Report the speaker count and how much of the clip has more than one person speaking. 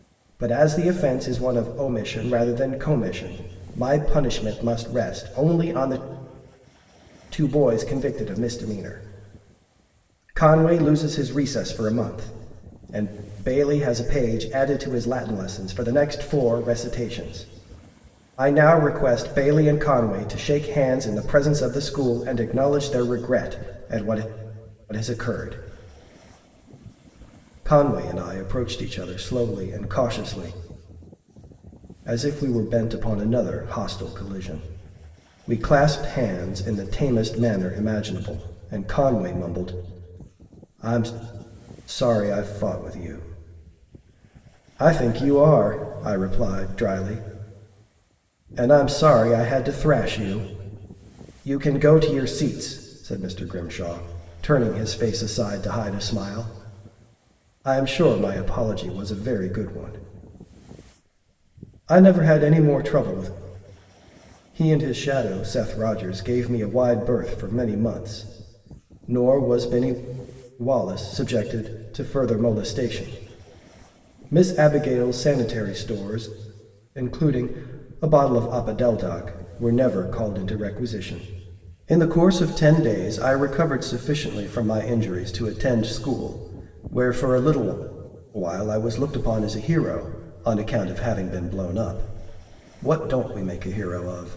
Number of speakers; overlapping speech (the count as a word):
one, no overlap